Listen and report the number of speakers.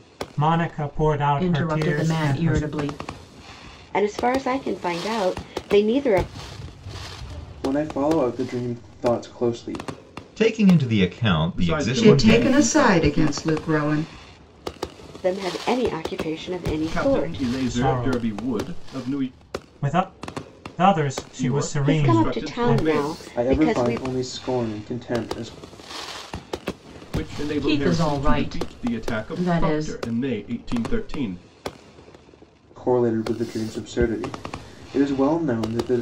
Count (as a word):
seven